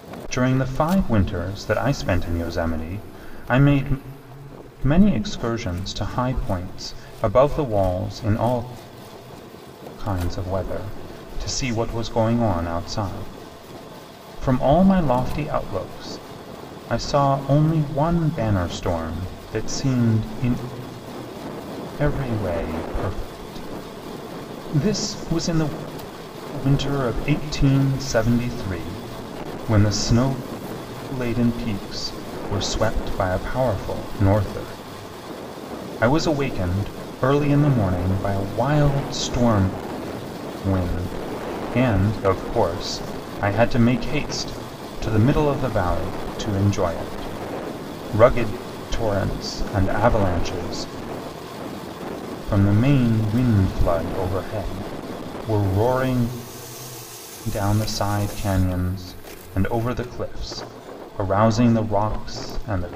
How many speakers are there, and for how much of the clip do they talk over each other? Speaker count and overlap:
one, no overlap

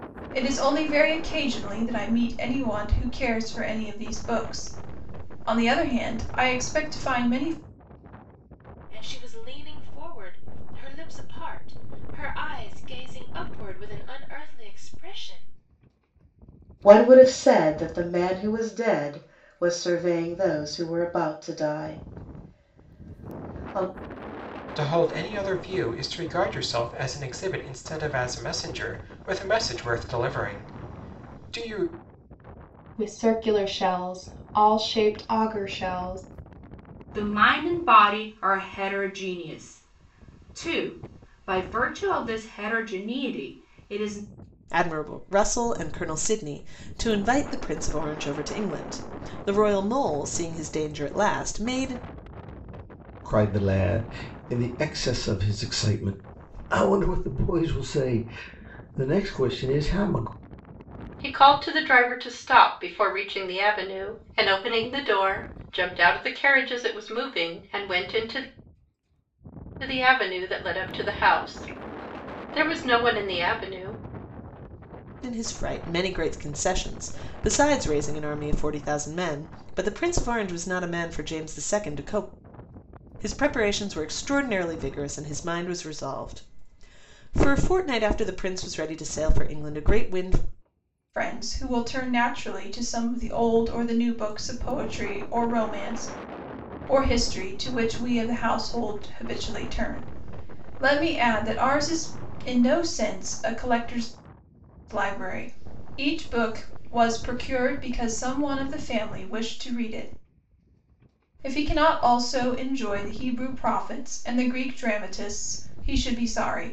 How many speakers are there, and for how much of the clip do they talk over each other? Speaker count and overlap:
nine, no overlap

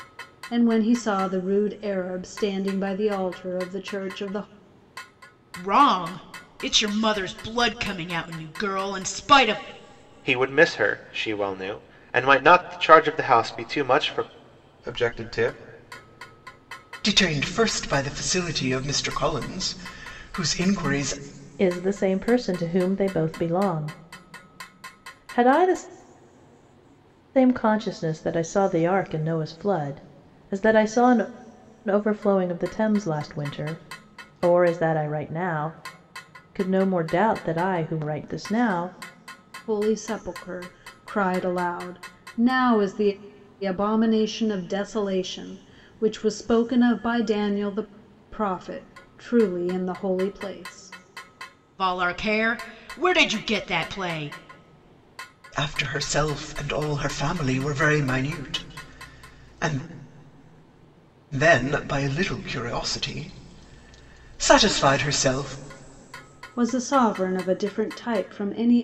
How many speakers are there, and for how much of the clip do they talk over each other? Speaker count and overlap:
six, no overlap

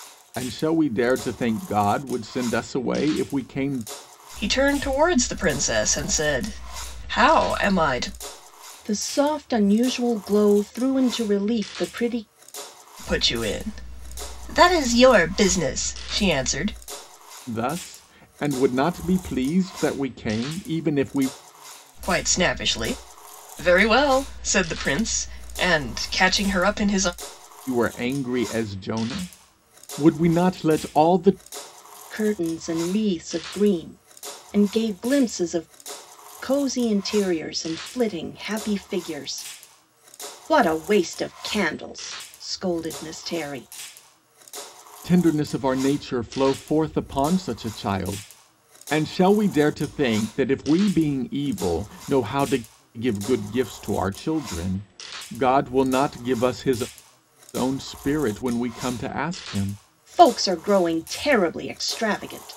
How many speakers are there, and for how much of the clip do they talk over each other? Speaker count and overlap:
three, no overlap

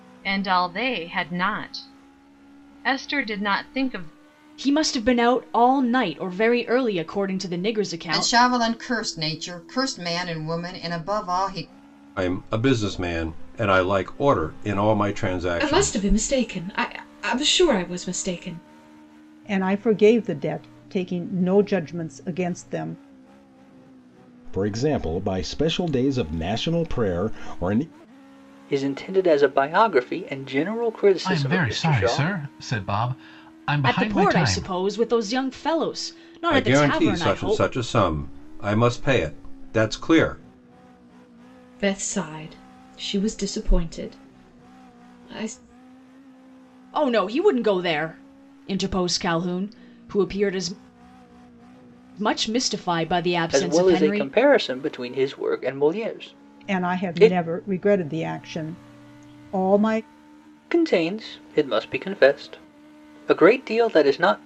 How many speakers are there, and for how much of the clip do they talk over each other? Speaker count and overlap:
nine, about 9%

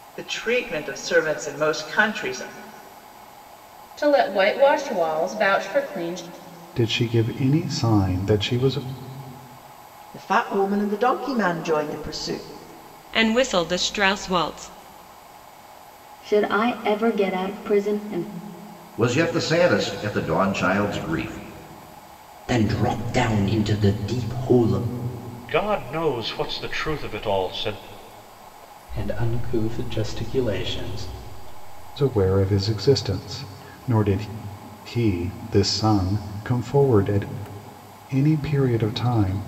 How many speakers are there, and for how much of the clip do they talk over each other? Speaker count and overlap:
ten, no overlap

